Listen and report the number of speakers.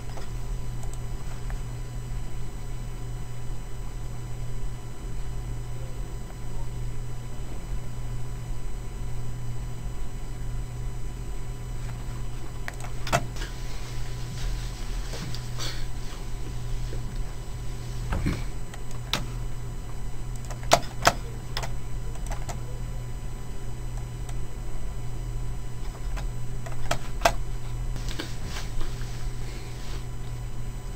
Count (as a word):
zero